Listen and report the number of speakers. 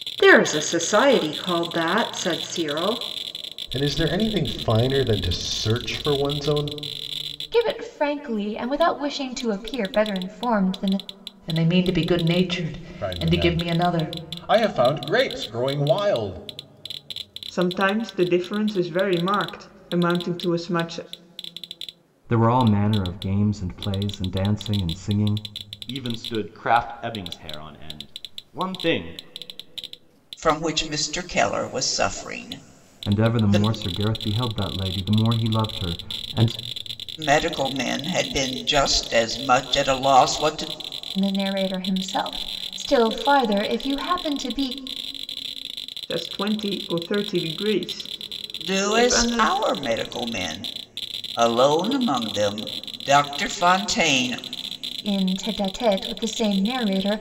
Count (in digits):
9